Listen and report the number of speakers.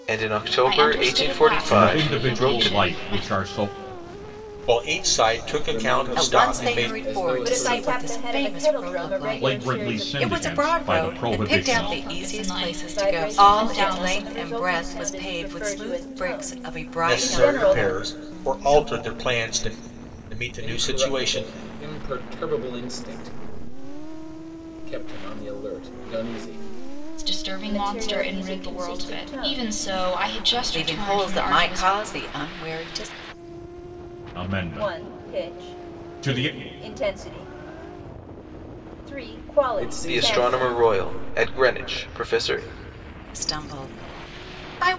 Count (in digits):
7